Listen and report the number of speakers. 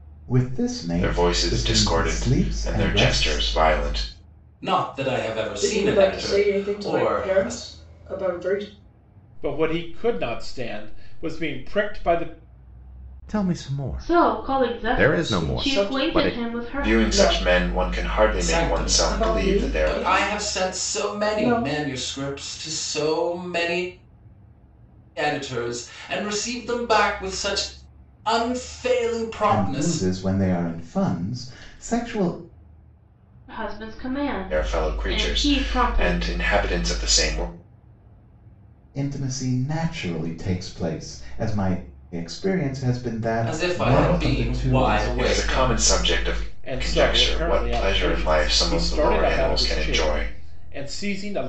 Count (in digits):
7